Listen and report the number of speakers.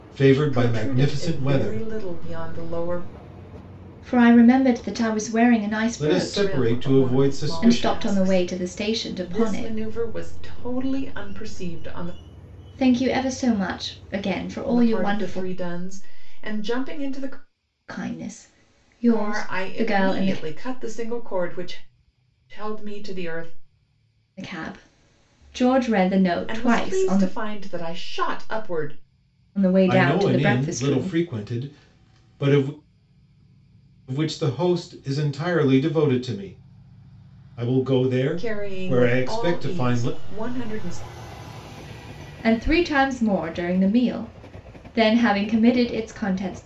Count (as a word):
three